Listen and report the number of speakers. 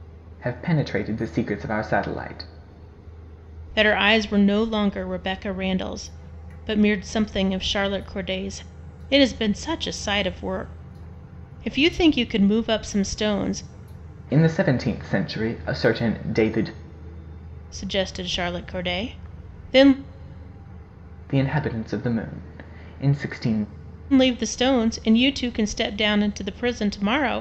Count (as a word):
two